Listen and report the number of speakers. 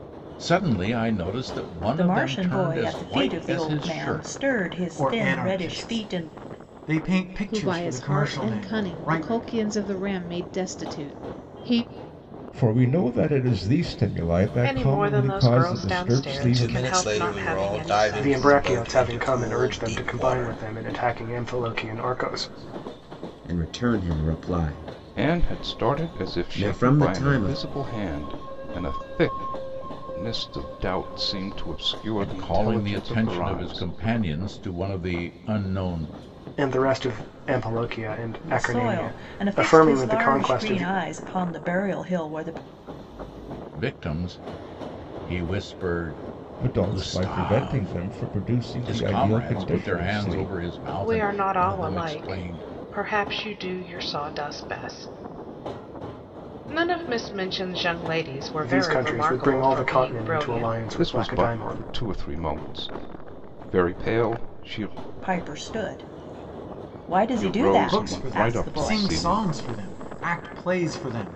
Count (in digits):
10